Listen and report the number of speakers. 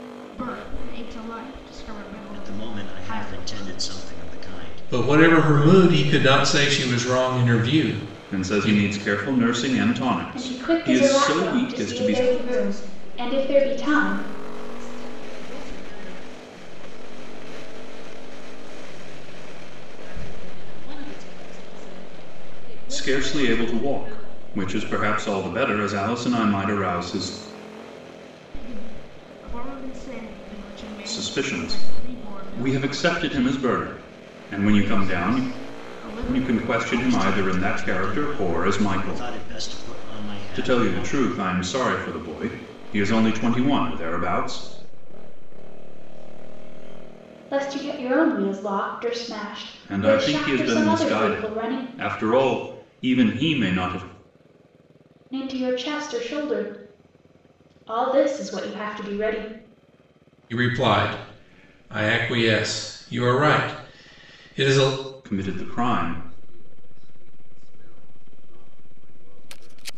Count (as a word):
seven